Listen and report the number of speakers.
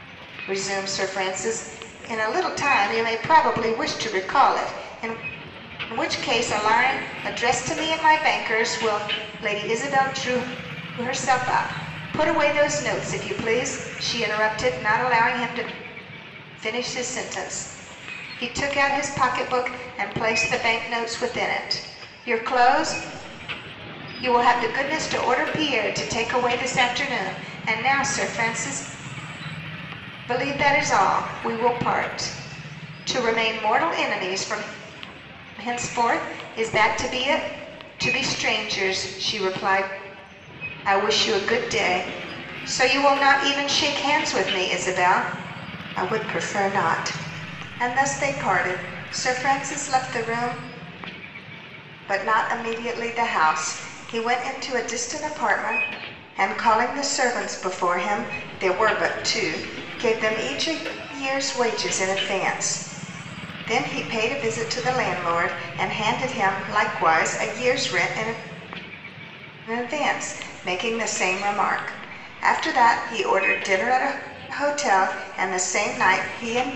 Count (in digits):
1